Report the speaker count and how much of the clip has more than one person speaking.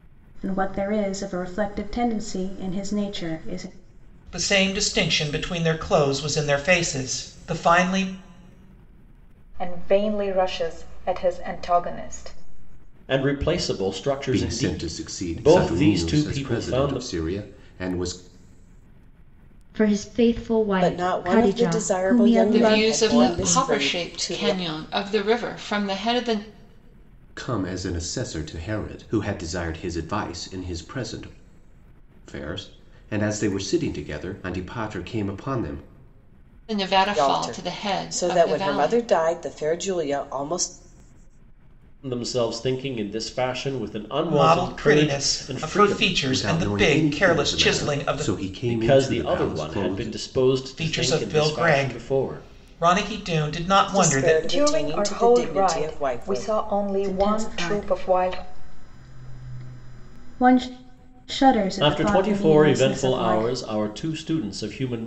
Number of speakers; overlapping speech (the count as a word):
eight, about 33%